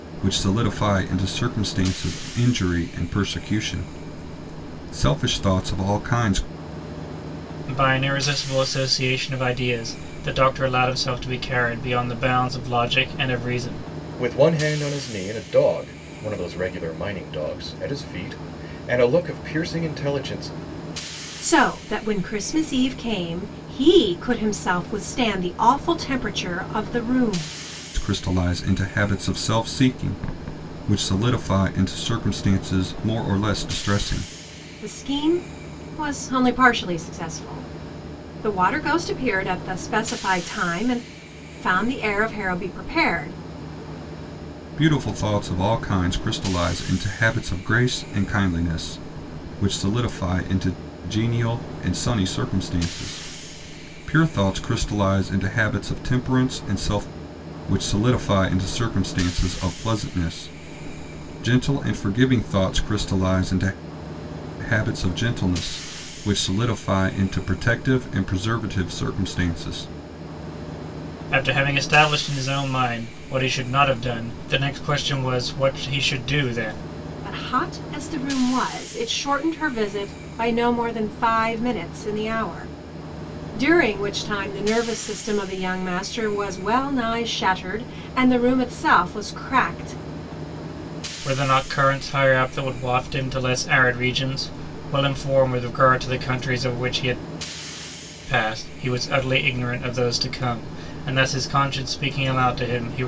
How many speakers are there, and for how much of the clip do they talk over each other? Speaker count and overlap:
four, no overlap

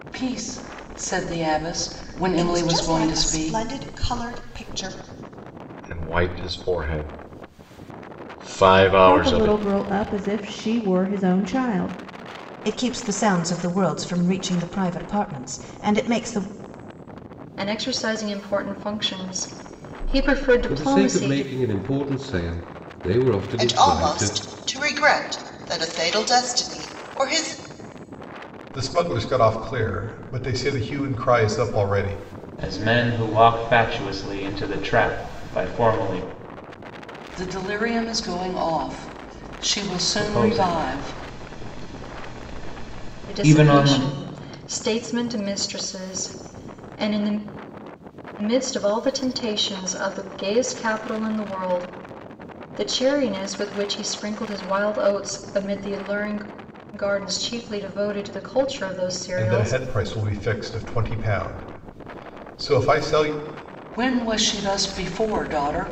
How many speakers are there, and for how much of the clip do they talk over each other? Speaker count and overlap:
ten, about 9%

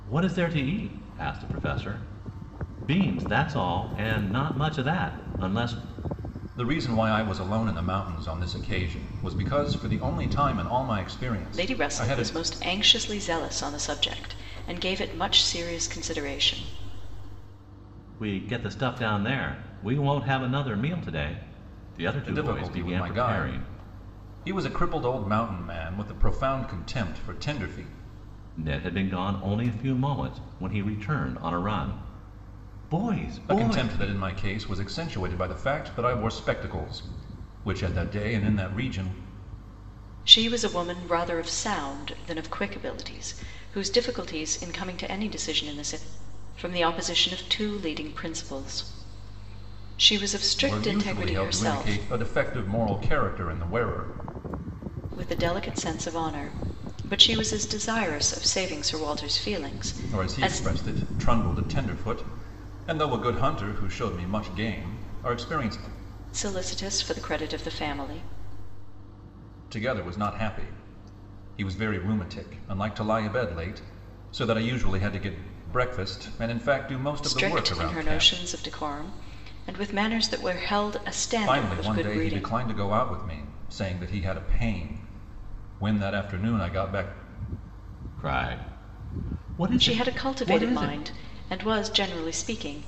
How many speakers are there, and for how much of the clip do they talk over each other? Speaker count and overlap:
three, about 9%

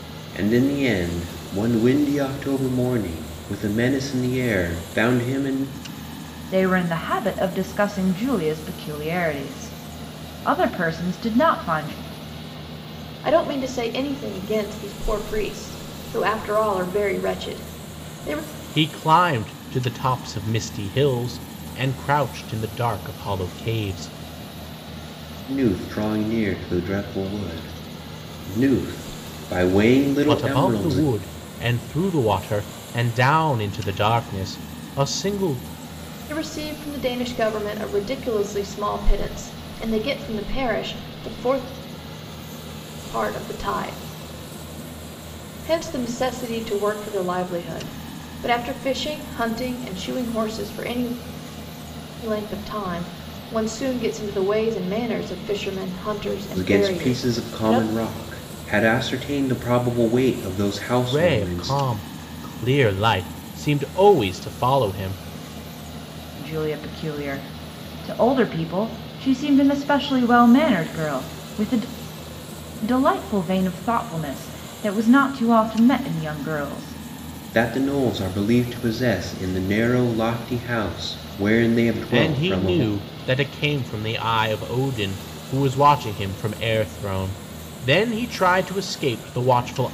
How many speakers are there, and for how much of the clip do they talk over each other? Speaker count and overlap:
four, about 4%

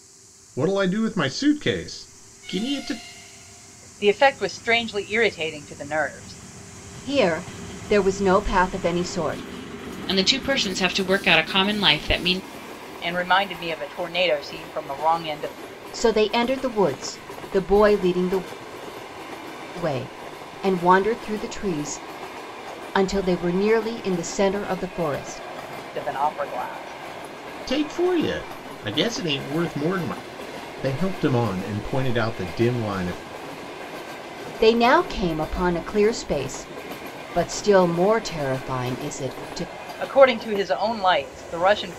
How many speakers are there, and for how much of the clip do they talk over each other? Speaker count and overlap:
four, no overlap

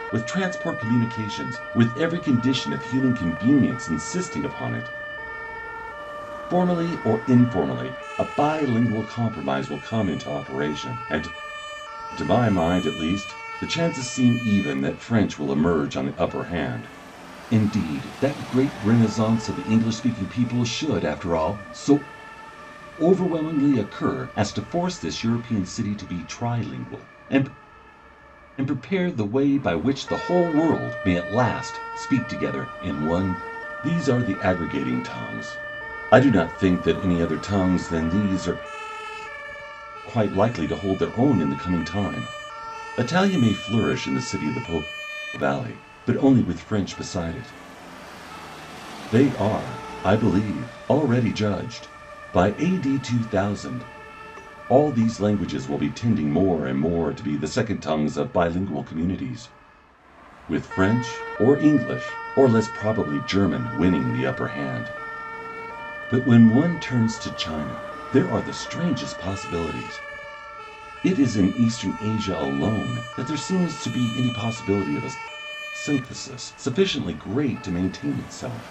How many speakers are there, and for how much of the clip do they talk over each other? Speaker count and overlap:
one, no overlap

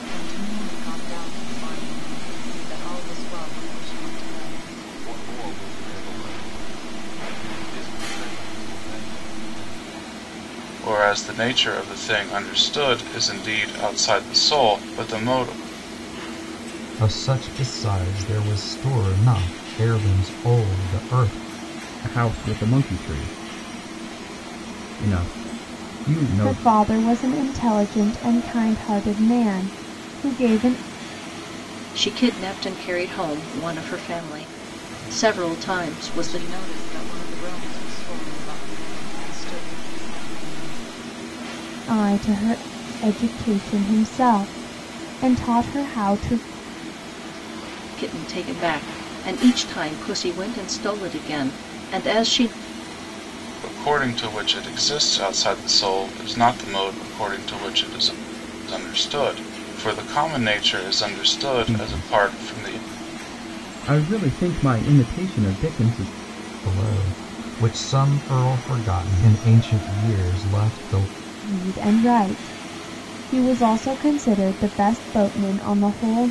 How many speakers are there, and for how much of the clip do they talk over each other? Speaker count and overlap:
seven, about 3%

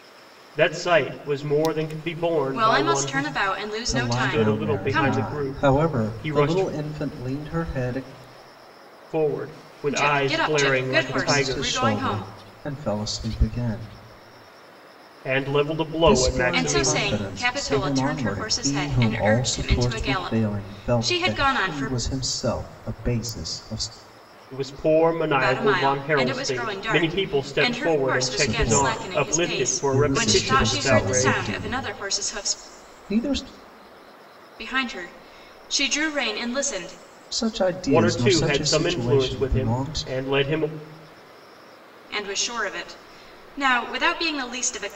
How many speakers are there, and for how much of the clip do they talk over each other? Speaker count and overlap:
three, about 48%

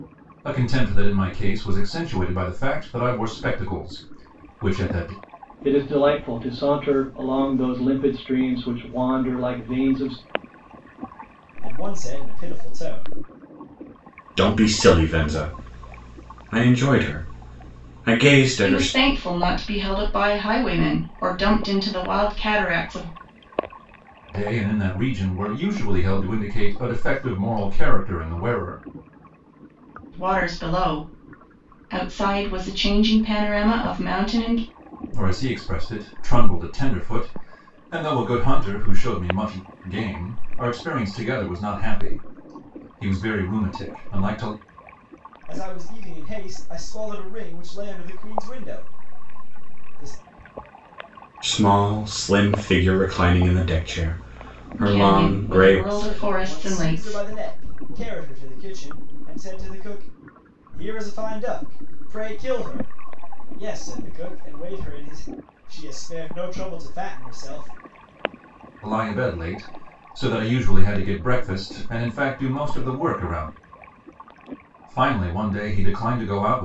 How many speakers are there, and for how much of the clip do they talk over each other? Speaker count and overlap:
five, about 4%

